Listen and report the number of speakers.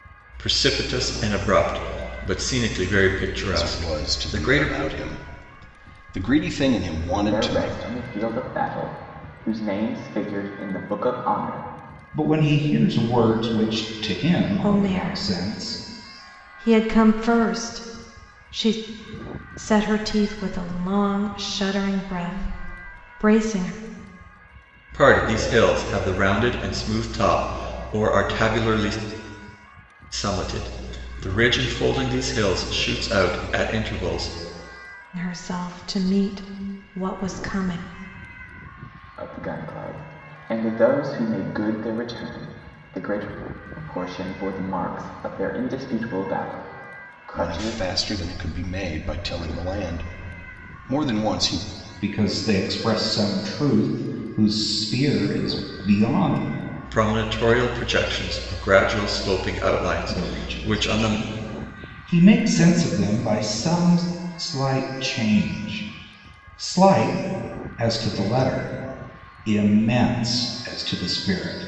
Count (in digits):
5